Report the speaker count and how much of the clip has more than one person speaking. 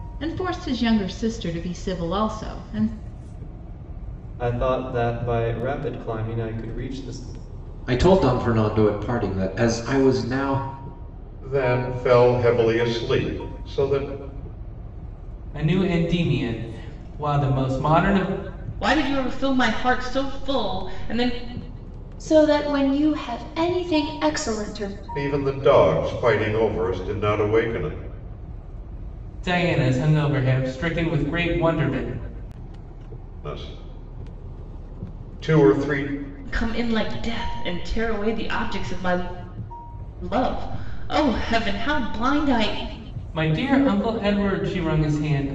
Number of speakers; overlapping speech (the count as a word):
seven, no overlap